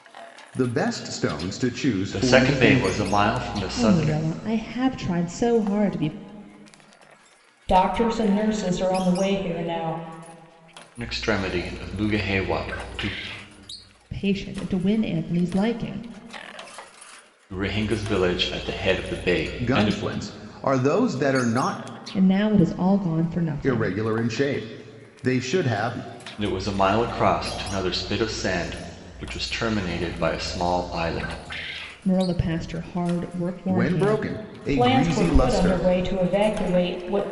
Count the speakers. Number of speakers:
4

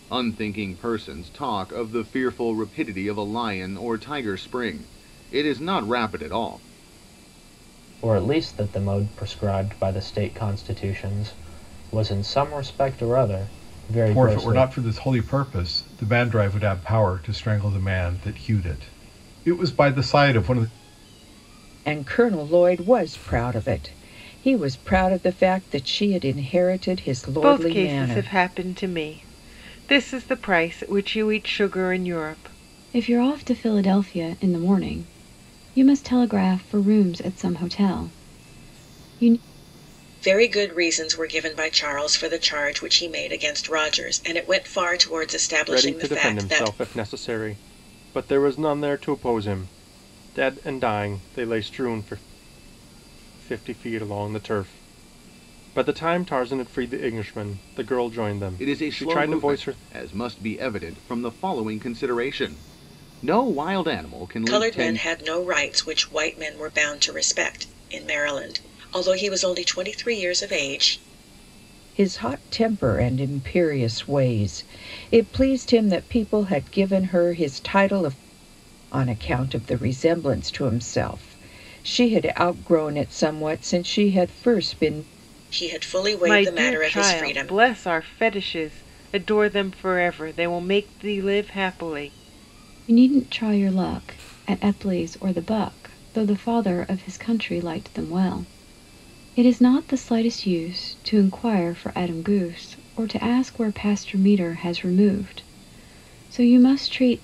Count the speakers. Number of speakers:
8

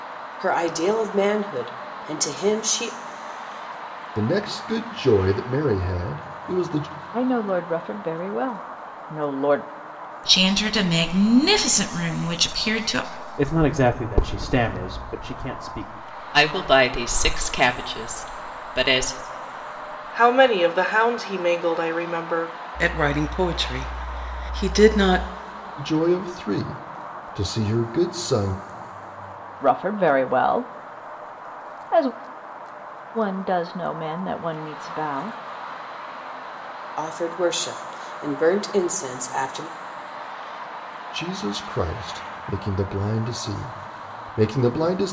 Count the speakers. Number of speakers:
8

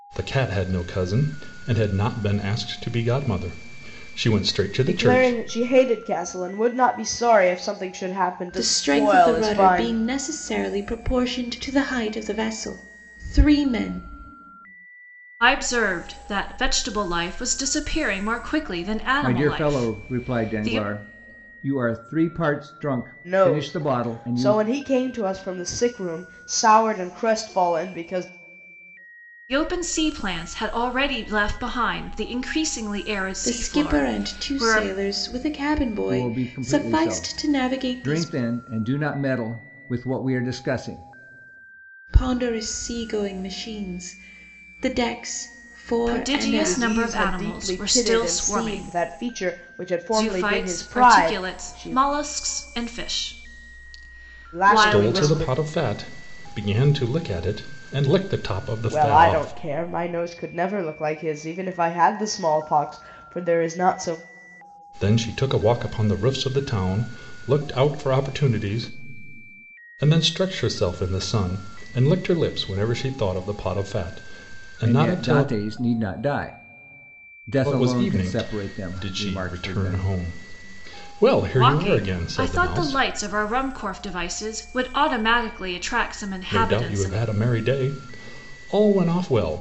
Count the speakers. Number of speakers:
5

